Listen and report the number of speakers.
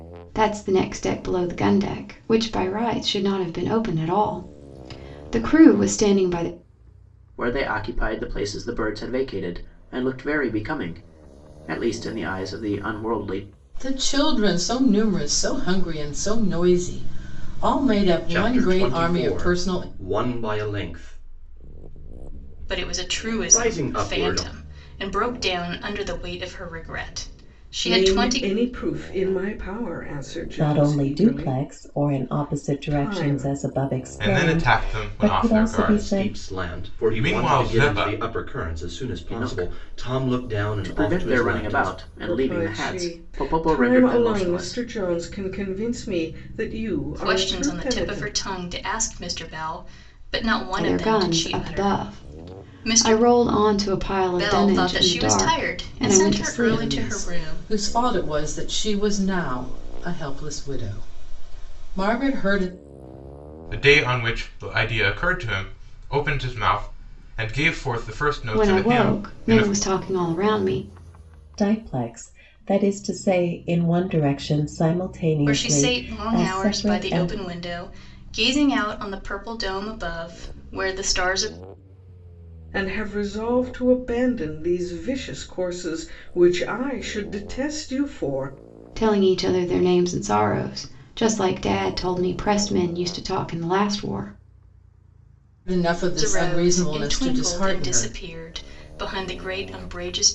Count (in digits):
8